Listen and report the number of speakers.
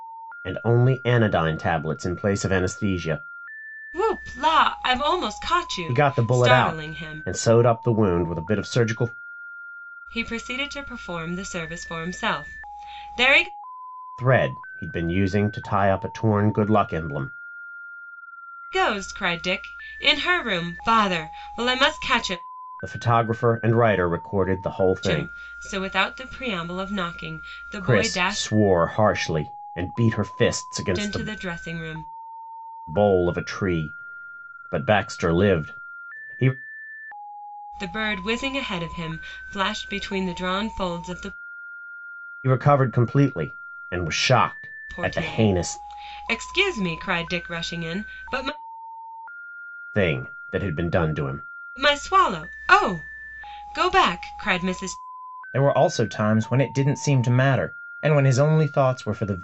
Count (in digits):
2